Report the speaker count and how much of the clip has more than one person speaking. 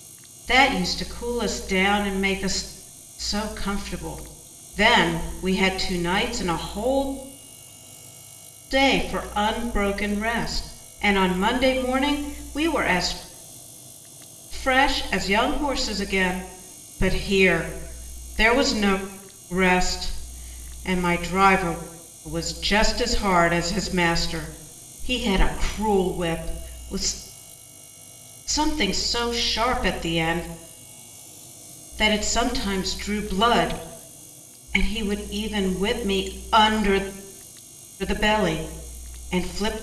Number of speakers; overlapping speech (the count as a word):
one, no overlap